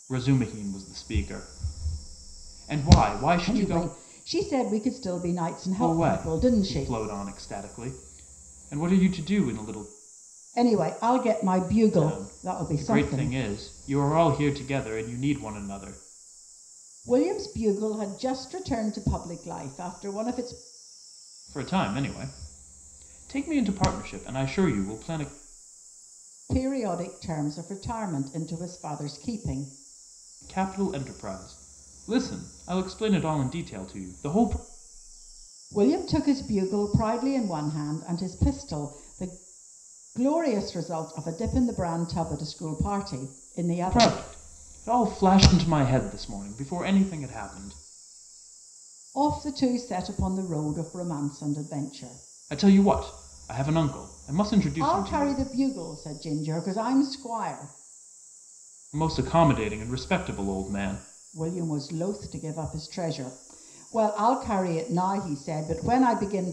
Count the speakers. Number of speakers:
two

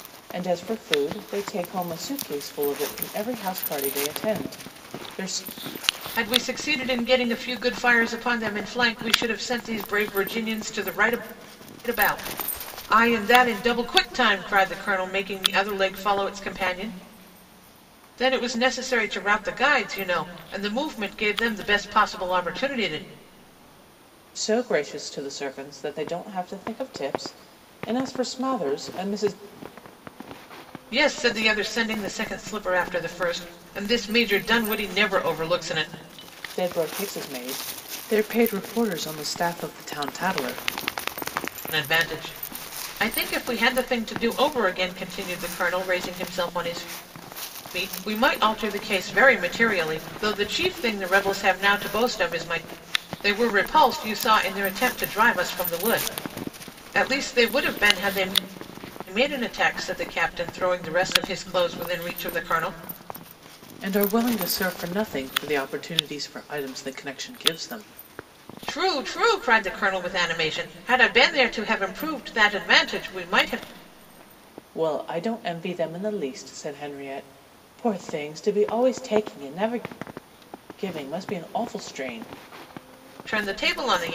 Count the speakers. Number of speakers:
two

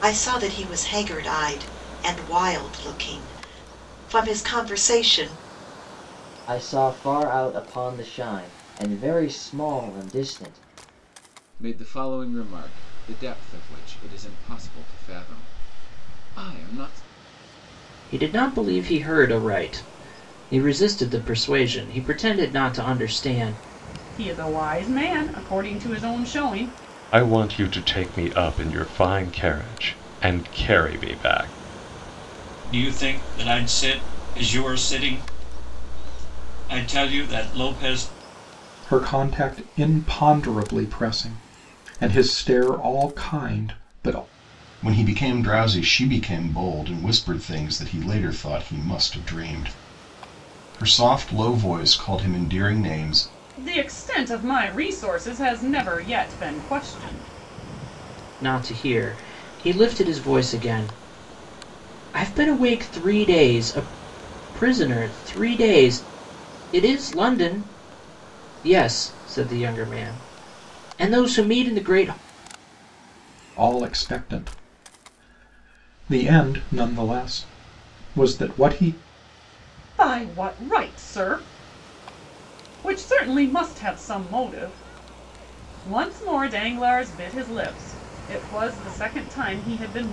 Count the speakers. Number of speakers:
nine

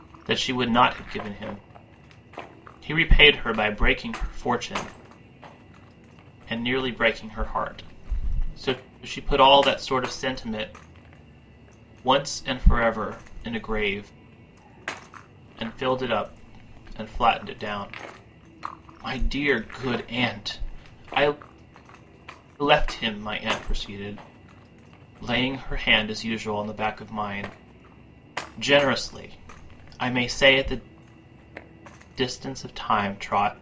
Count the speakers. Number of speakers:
one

